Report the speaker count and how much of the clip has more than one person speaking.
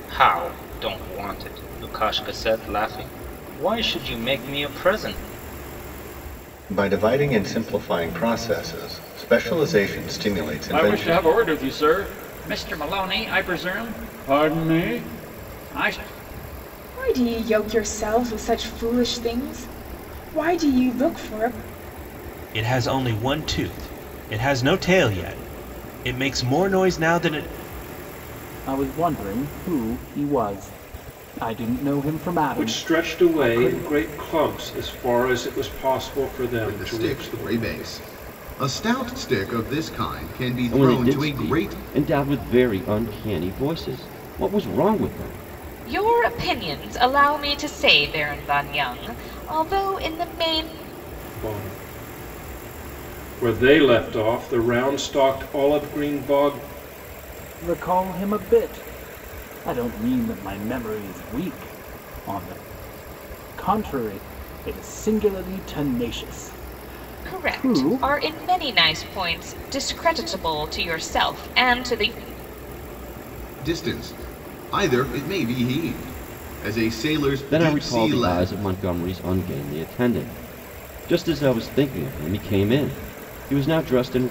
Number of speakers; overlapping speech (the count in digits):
10, about 7%